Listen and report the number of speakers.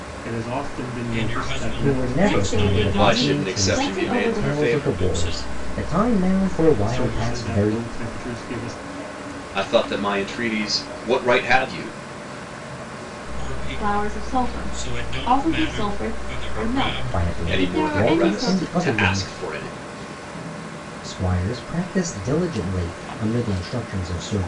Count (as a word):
five